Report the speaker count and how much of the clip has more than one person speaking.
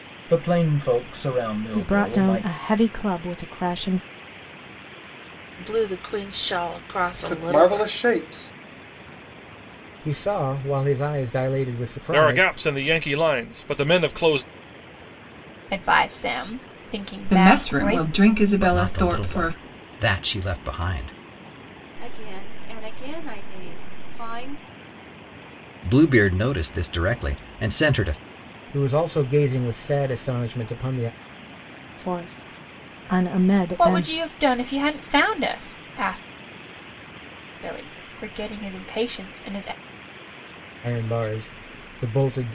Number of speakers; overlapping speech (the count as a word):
ten, about 11%